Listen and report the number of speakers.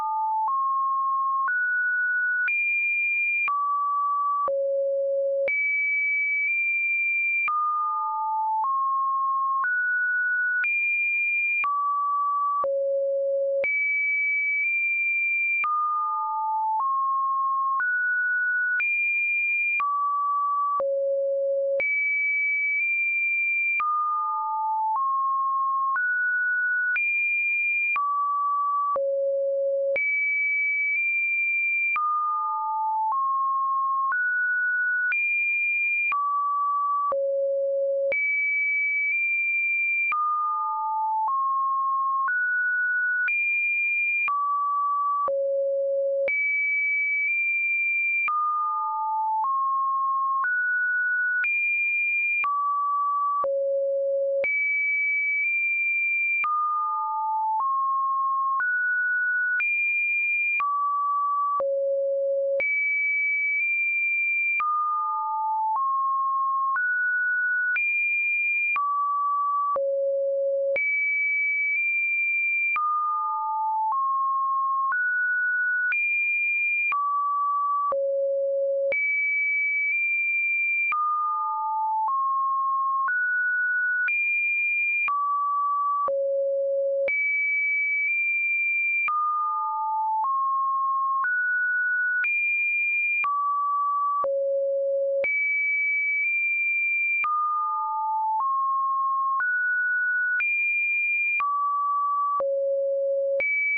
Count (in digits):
0